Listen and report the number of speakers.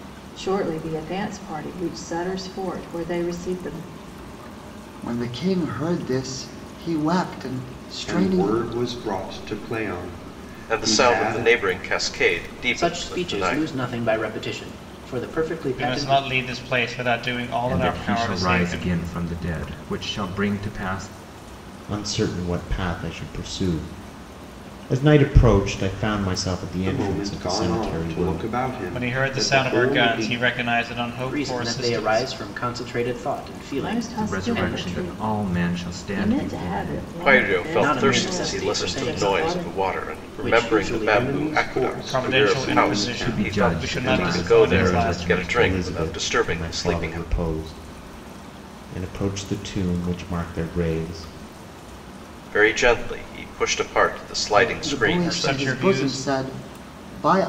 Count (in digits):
8